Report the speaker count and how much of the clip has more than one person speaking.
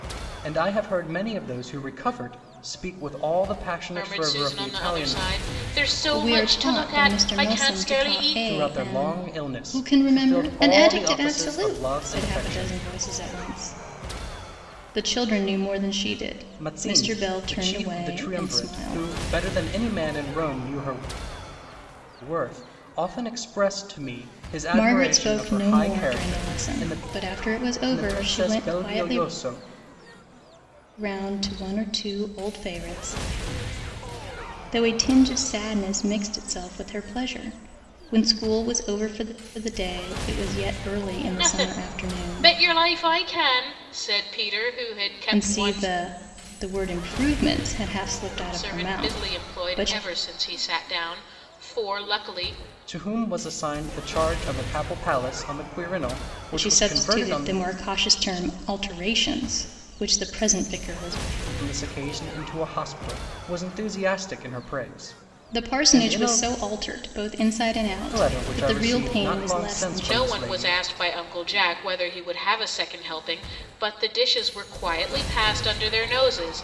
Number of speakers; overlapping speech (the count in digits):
3, about 29%